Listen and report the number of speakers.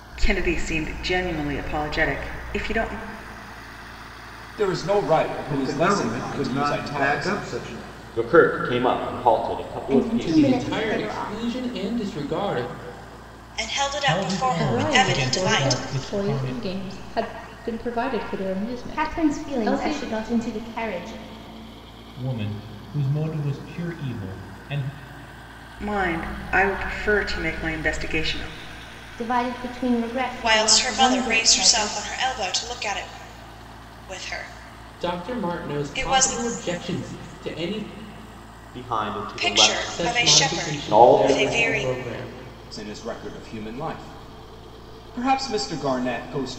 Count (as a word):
nine